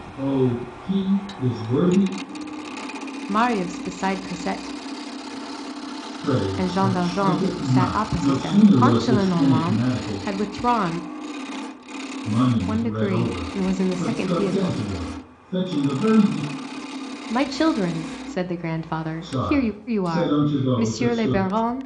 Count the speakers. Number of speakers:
two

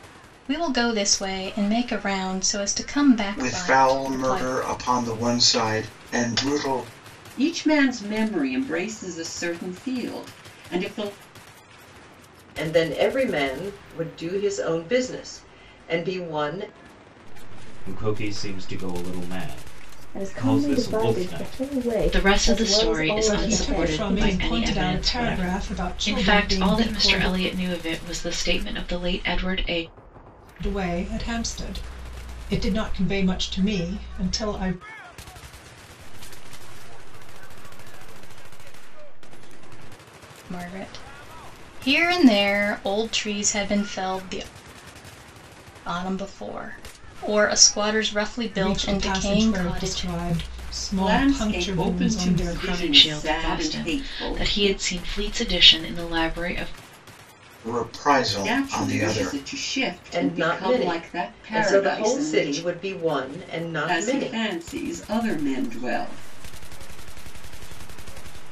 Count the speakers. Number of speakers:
nine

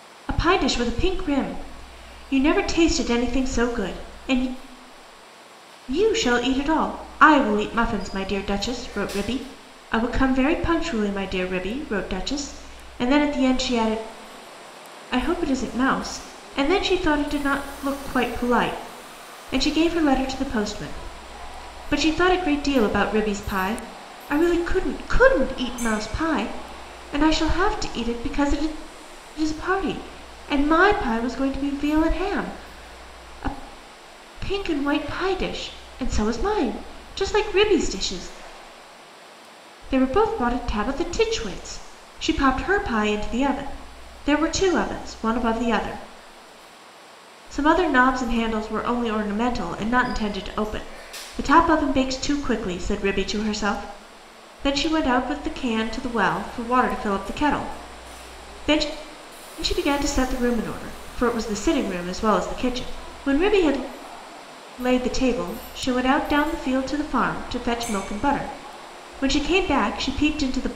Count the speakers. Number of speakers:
one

